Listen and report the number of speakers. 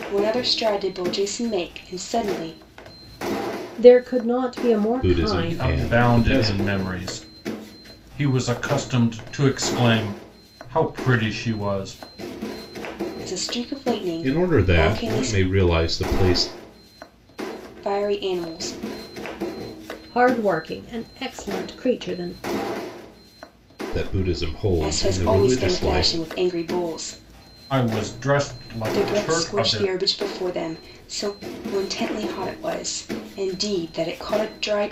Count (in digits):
4